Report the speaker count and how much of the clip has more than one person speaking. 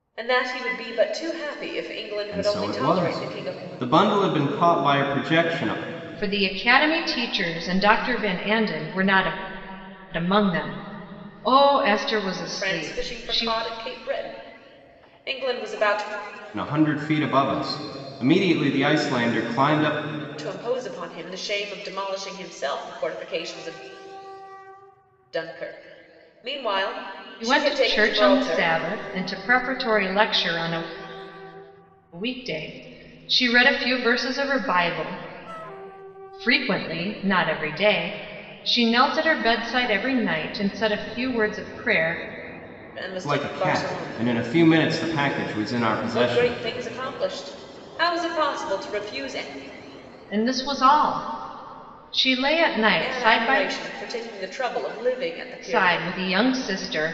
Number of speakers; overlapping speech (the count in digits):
3, about 11%